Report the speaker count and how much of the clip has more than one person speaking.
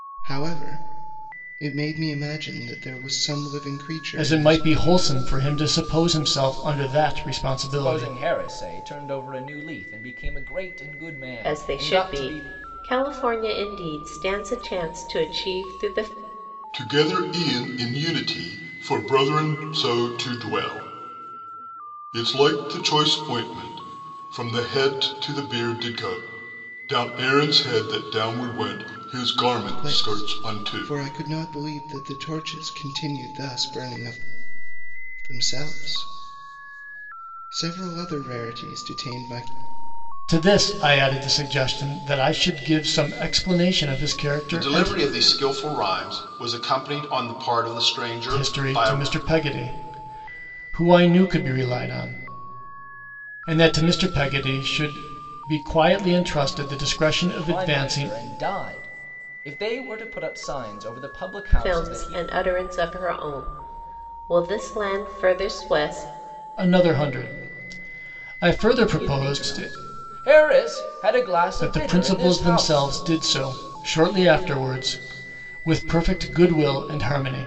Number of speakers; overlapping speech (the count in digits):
5, about 11%